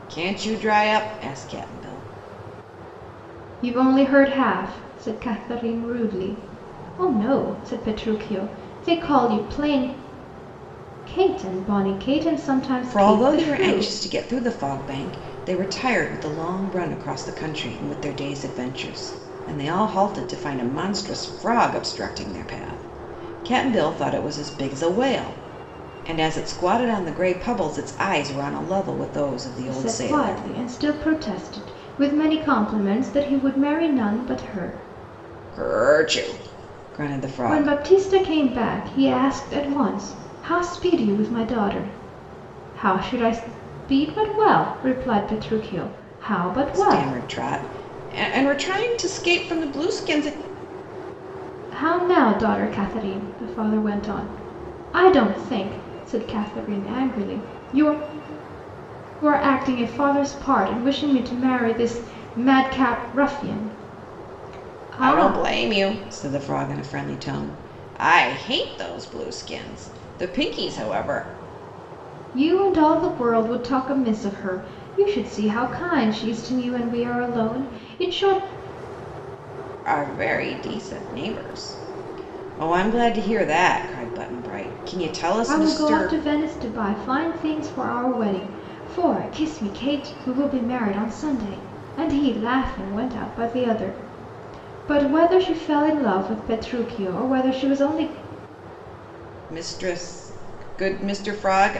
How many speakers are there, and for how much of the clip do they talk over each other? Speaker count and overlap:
two, about 4%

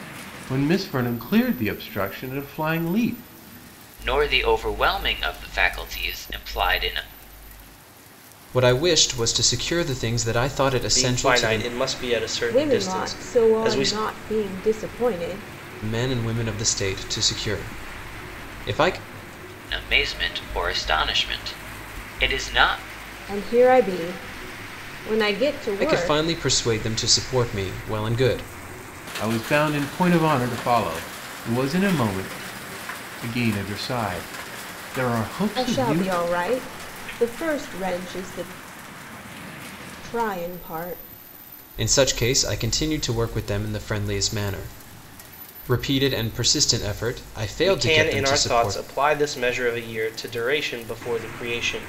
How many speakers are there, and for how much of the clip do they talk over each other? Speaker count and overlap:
five, about 9%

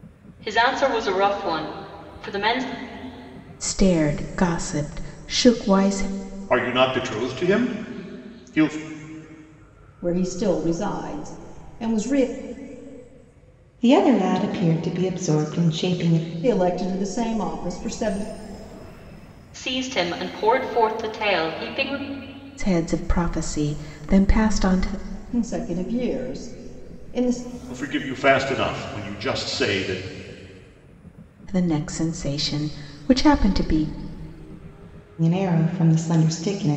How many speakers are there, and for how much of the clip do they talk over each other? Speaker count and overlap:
five, no overlap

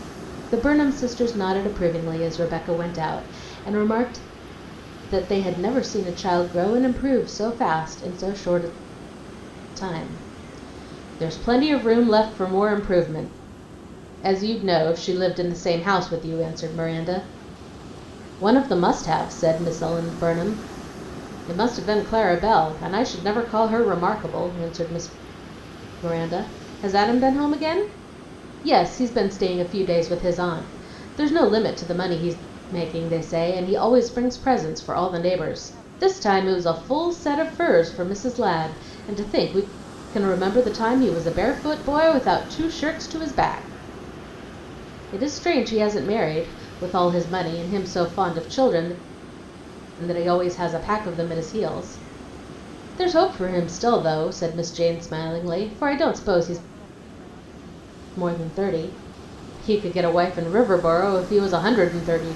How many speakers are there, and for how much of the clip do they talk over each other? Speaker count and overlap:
one, no overlap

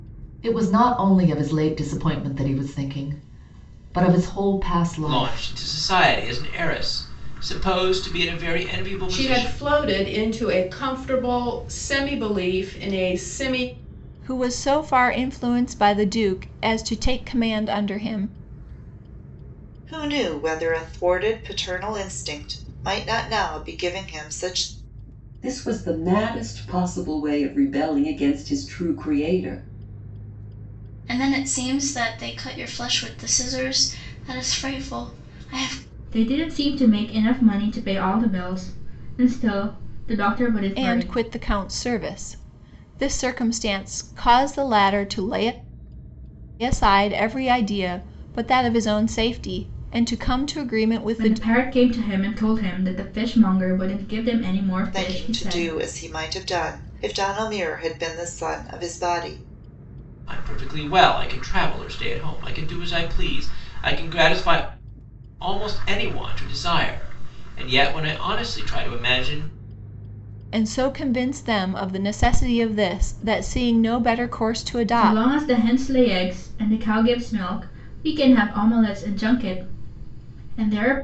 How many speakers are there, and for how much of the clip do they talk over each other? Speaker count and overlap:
eight, about 4%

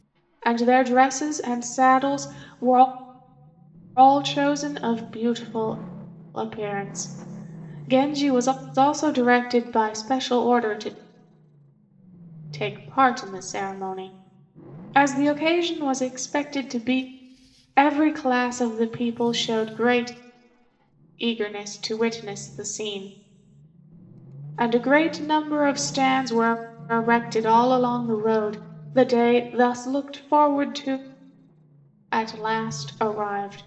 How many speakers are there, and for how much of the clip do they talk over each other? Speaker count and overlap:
one, no overlap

